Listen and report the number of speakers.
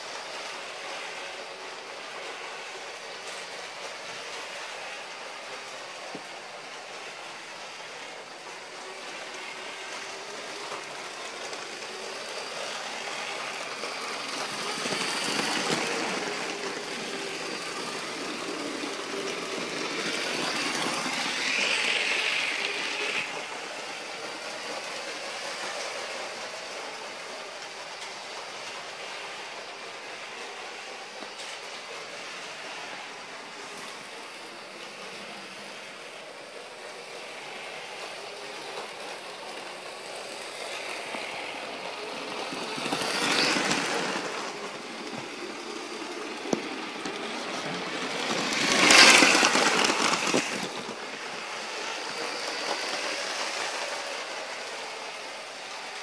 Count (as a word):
zero